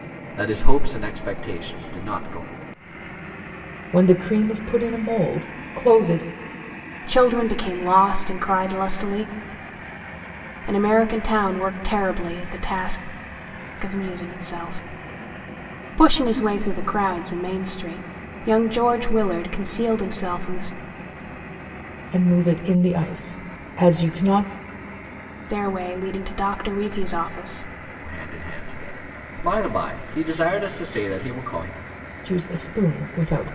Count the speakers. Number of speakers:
three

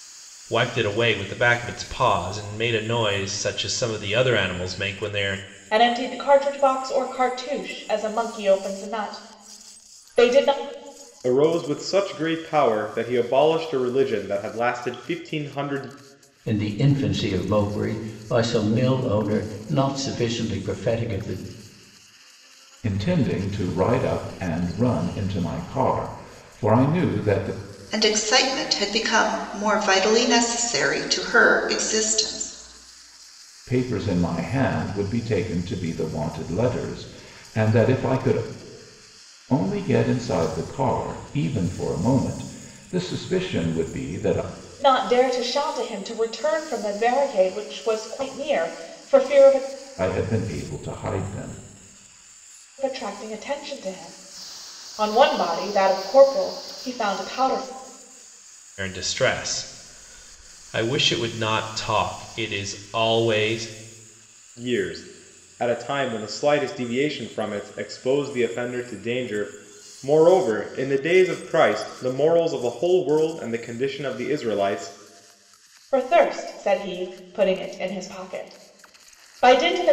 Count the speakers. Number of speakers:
six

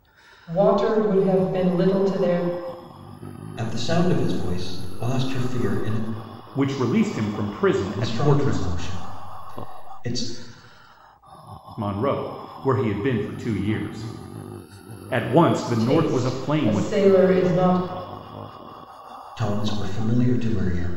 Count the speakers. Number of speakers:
three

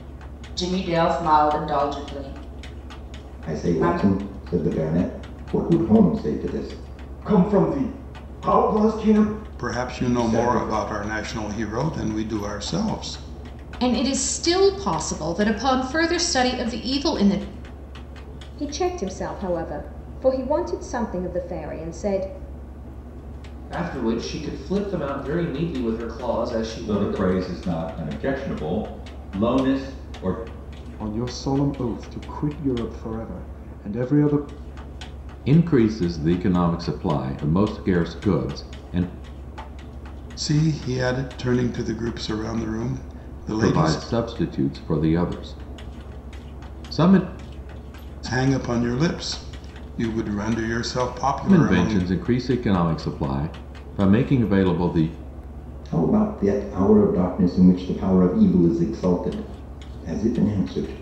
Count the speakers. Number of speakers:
ten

